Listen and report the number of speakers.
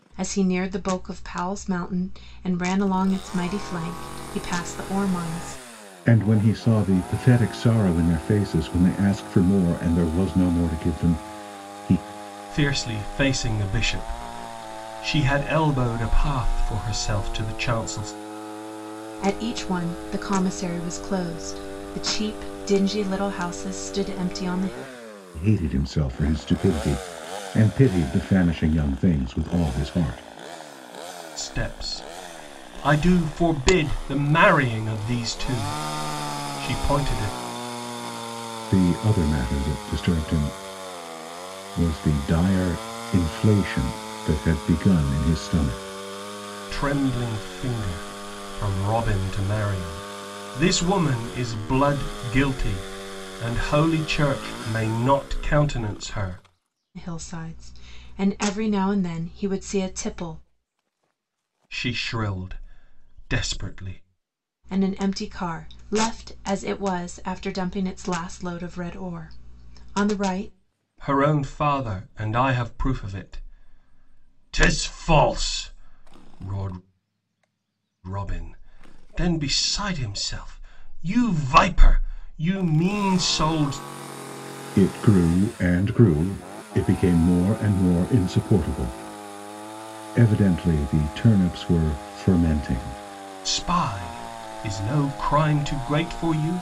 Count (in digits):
3